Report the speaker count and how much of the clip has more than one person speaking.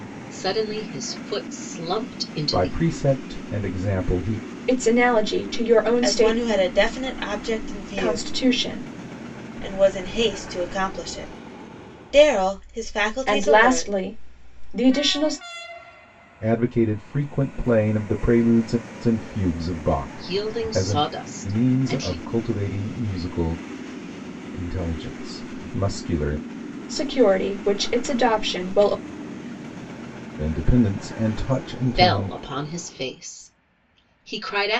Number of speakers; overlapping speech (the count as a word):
four, about 12%